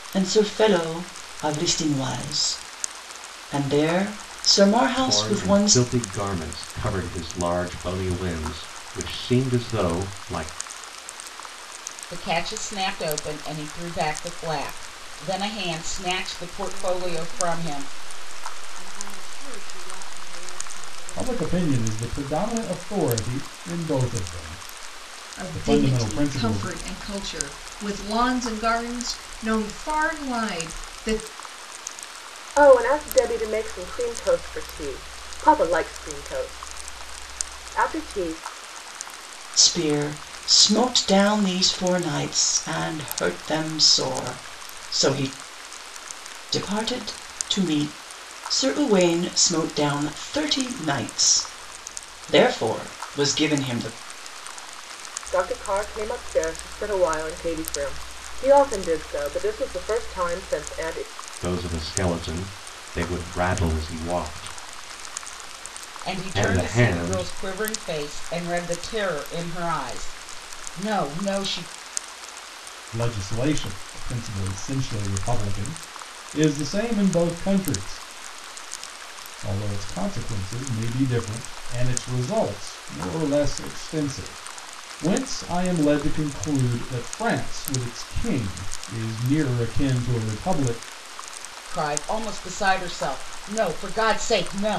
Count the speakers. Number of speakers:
seven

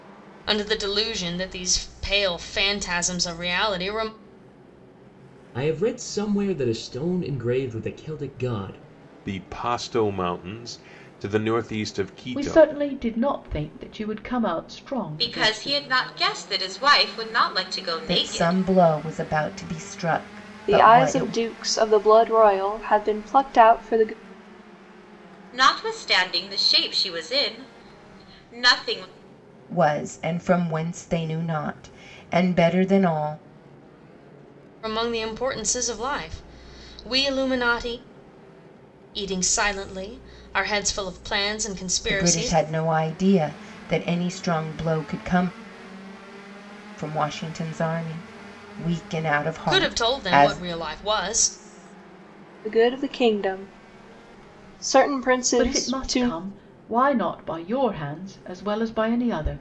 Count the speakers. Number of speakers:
seven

